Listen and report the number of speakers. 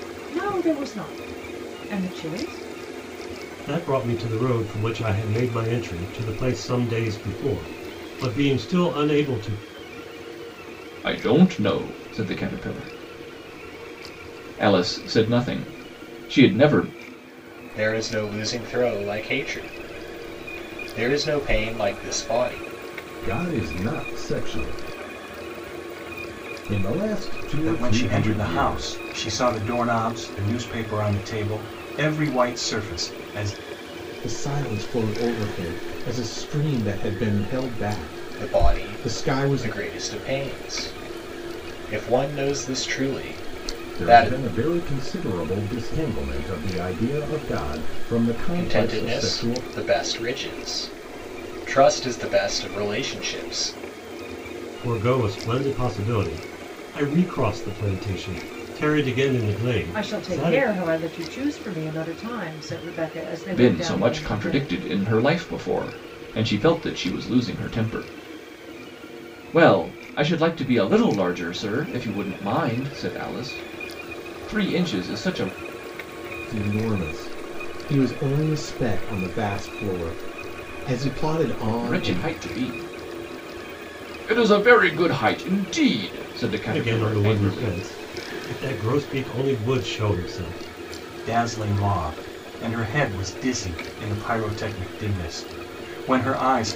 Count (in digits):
7